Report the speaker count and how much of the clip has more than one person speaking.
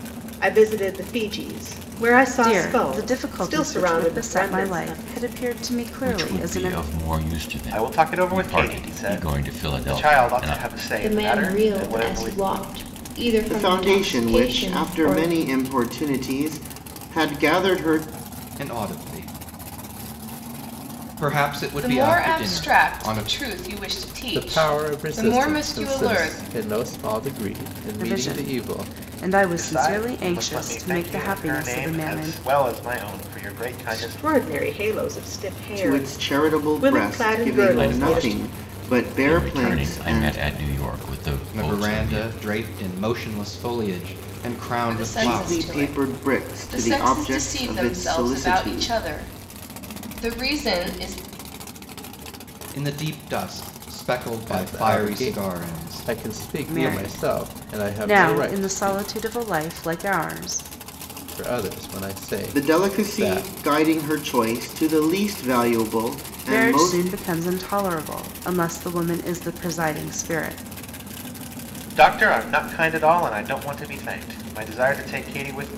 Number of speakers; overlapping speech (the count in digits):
9, about 43%